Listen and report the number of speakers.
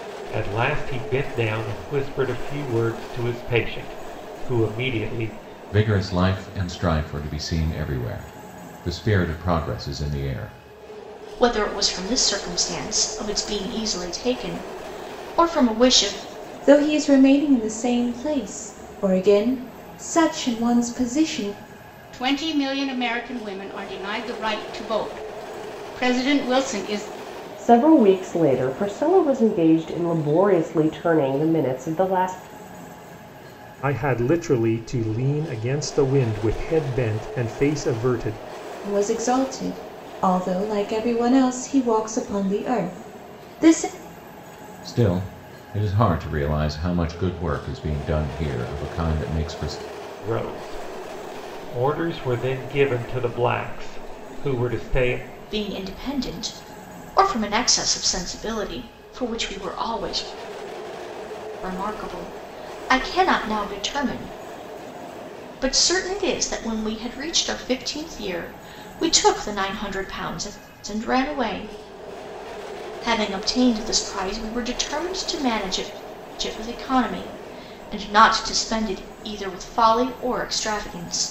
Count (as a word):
seven